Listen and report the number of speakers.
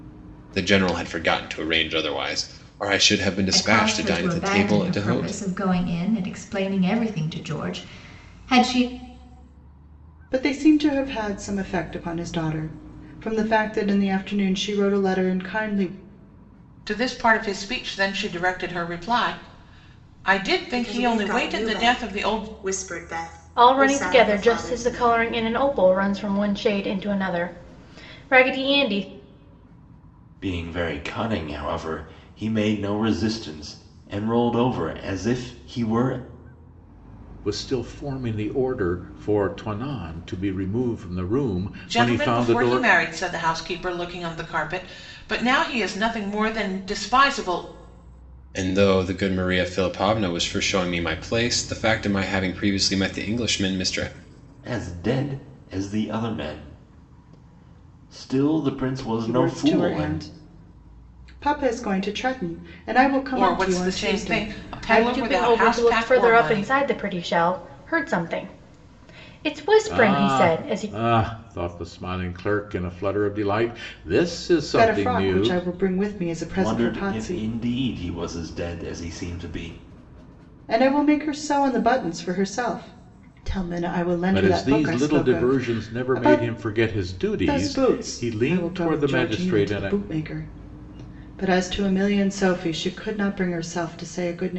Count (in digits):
8